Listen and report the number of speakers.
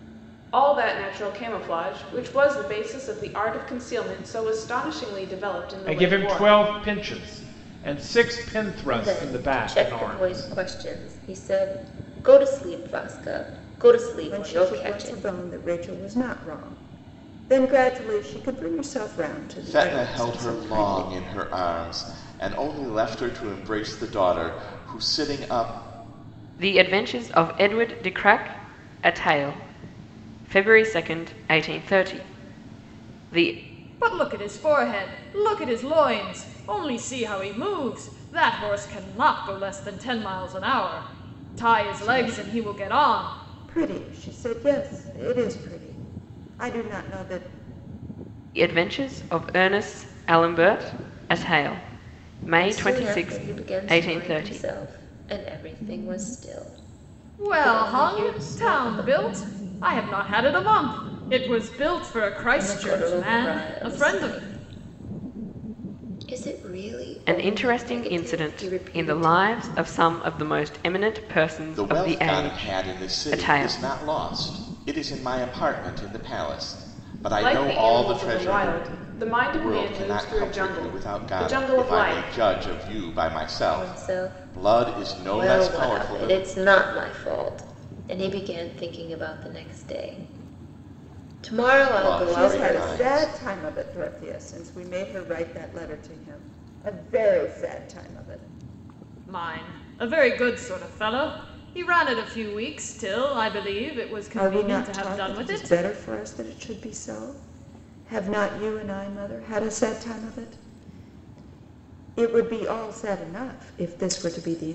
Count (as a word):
seven